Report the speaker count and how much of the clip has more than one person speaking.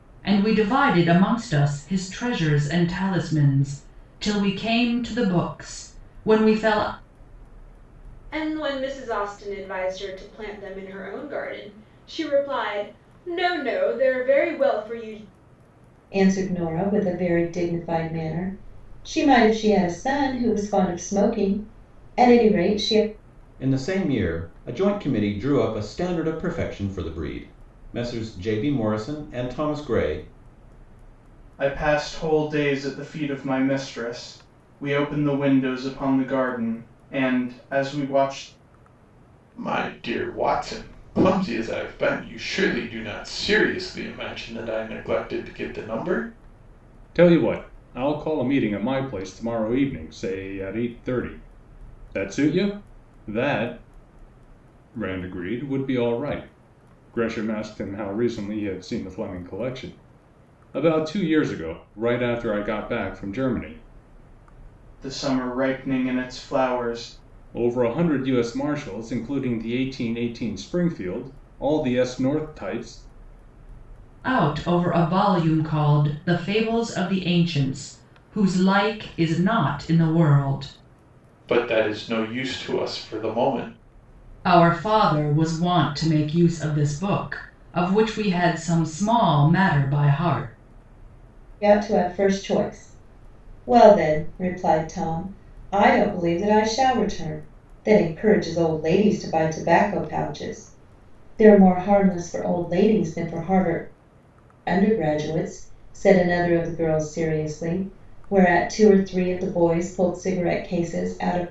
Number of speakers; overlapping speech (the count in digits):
7, no overlap